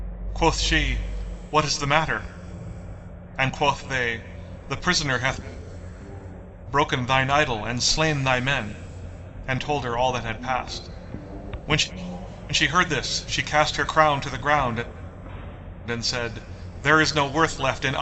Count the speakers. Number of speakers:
1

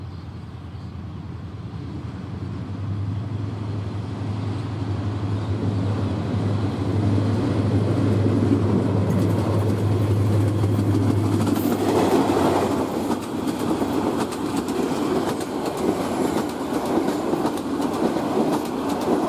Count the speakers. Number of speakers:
0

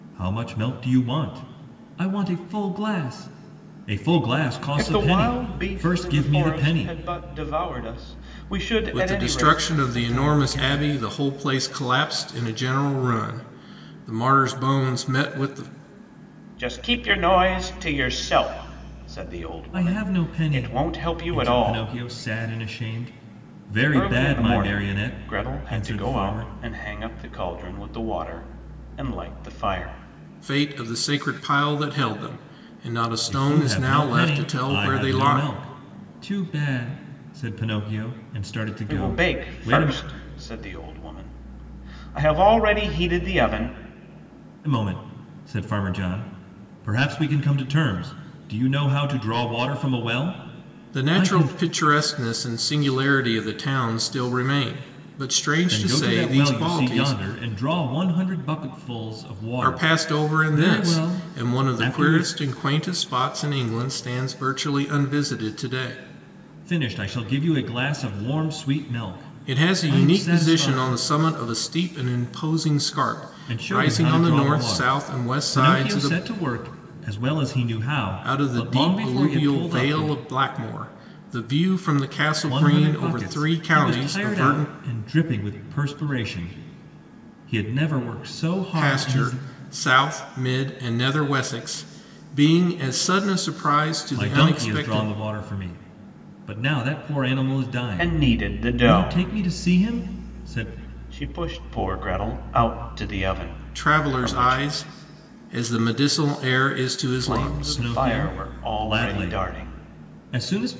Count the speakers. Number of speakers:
3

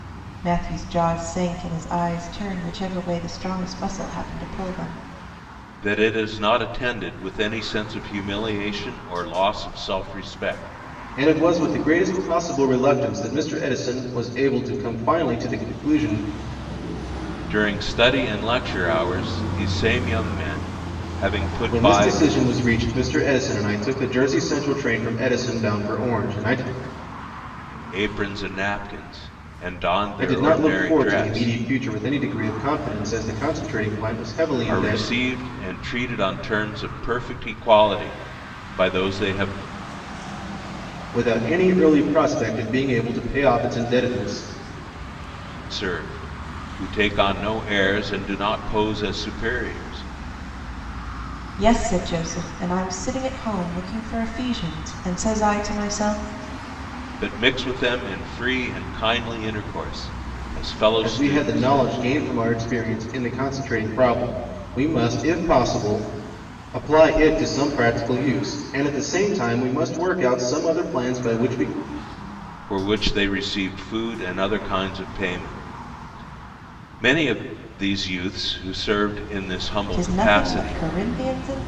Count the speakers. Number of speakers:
3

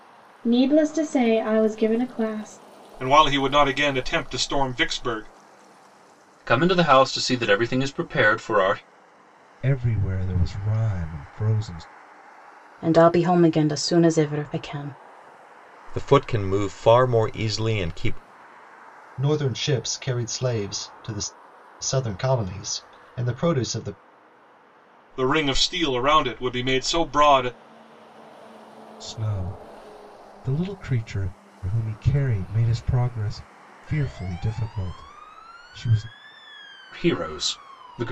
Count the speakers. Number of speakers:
7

